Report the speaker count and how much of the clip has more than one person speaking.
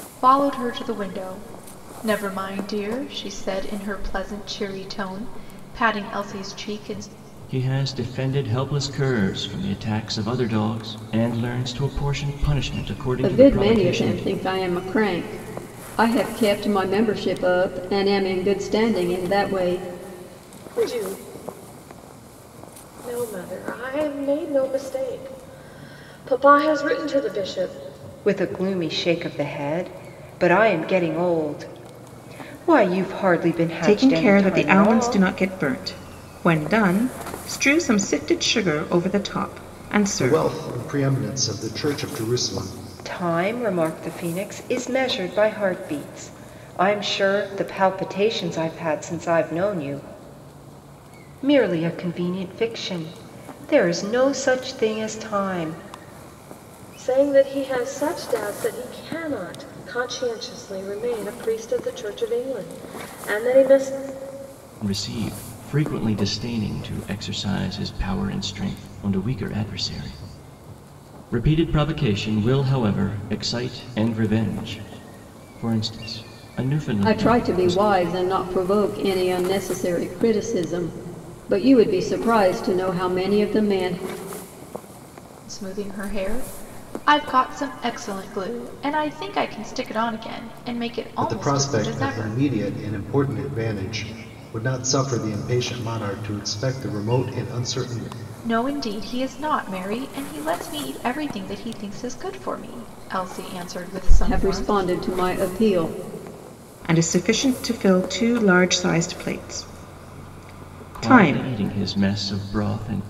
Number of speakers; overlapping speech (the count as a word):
seven, about 6%